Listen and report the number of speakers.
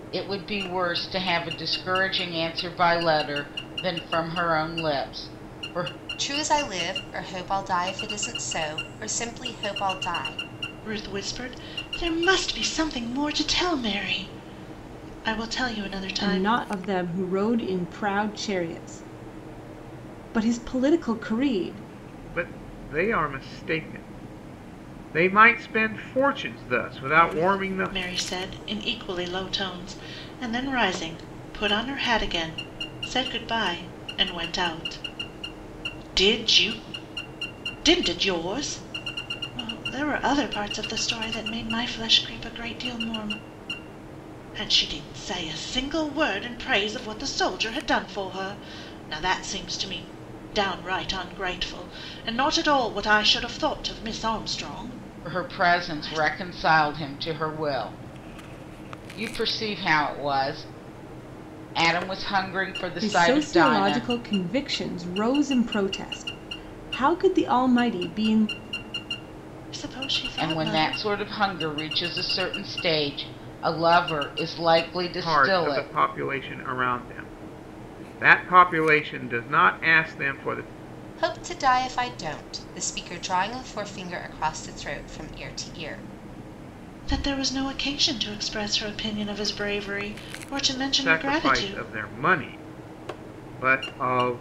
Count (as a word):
five